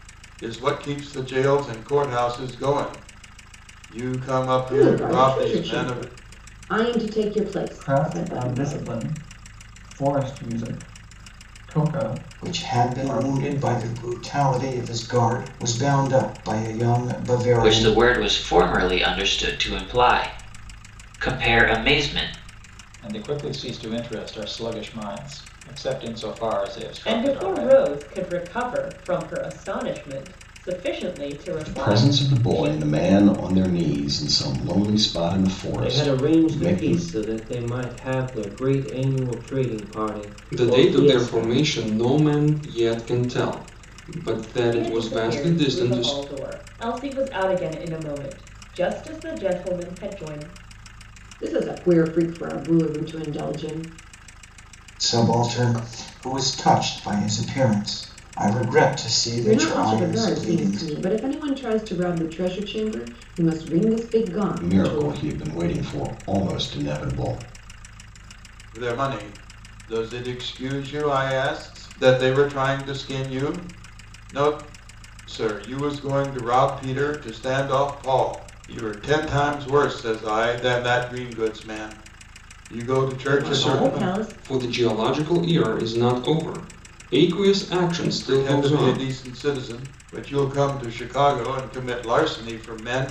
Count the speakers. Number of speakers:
10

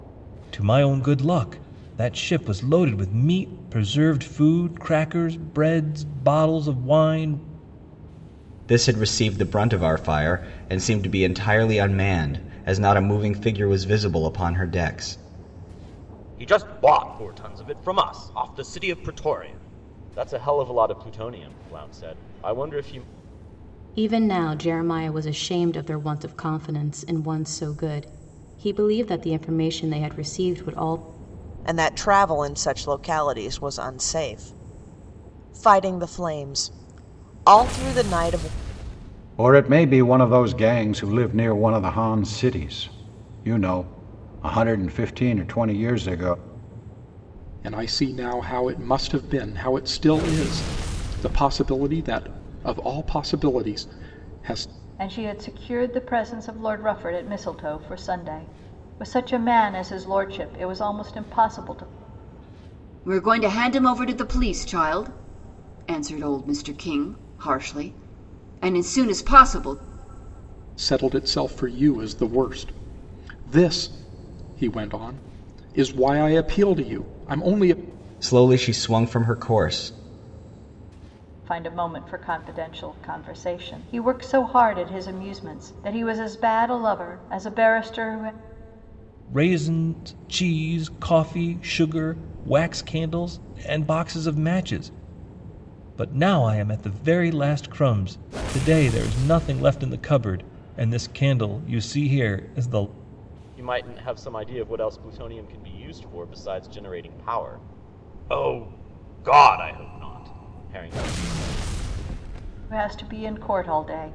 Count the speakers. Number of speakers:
9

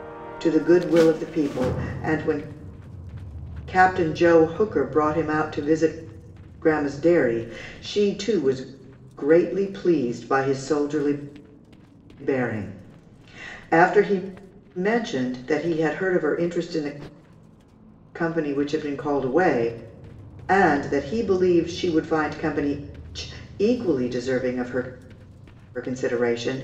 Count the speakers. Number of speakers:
1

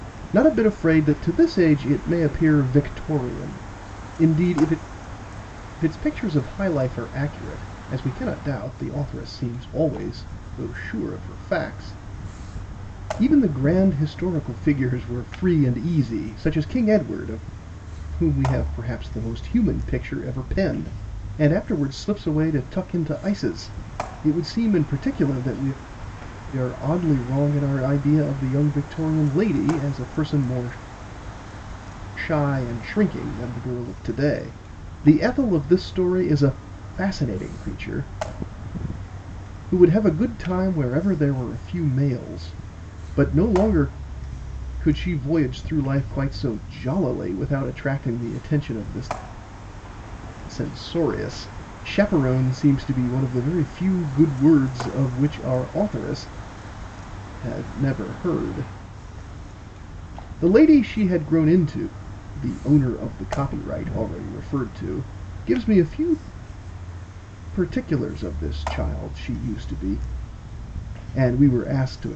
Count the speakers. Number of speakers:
1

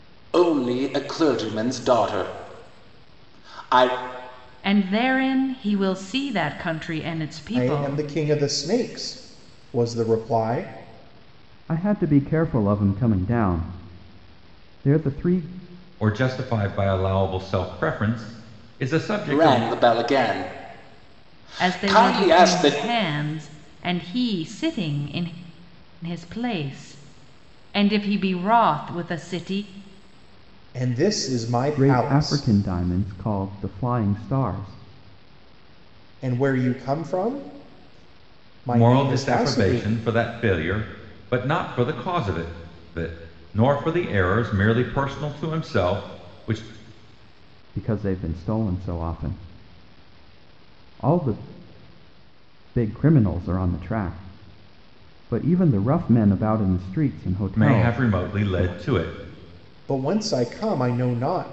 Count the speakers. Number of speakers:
5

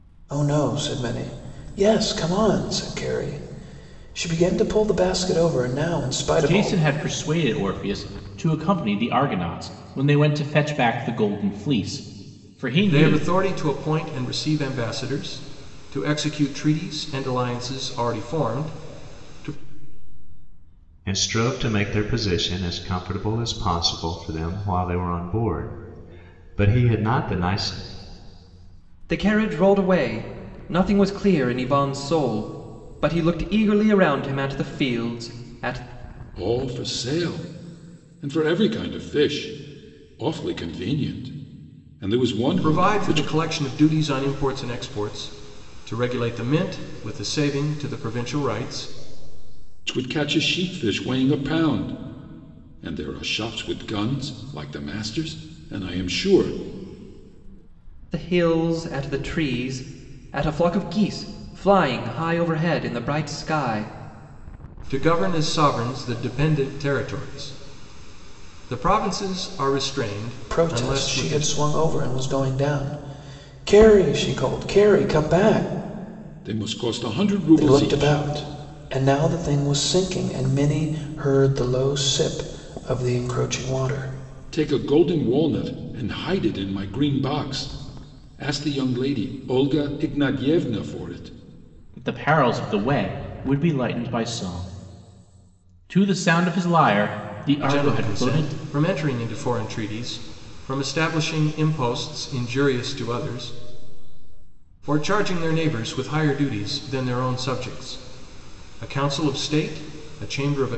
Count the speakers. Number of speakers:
6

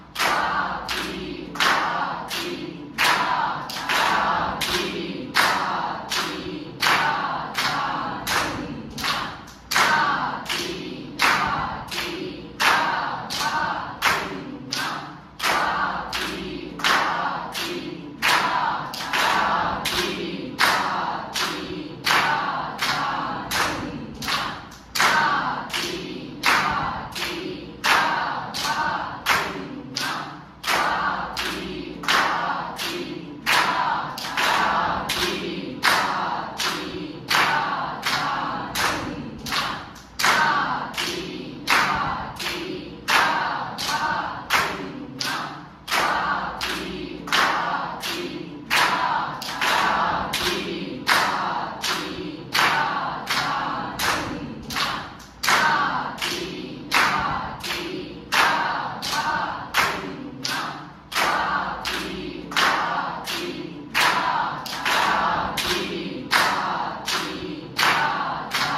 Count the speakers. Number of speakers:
0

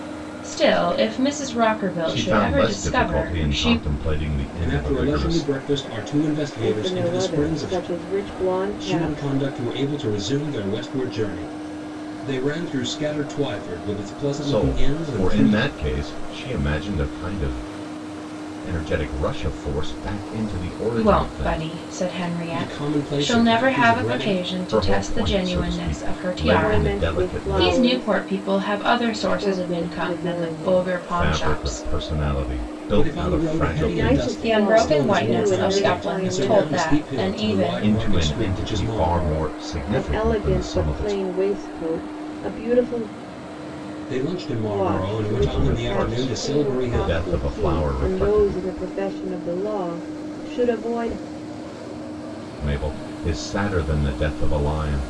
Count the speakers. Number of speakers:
4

